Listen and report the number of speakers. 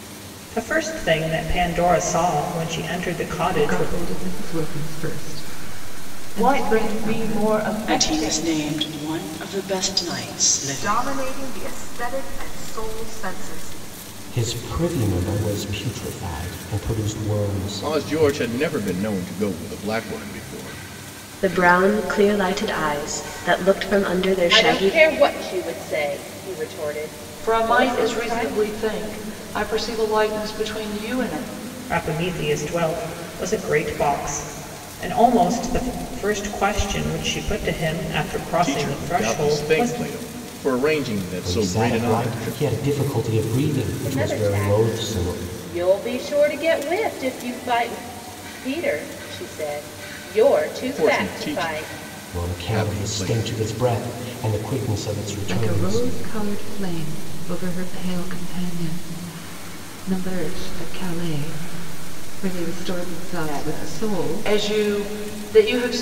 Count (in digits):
10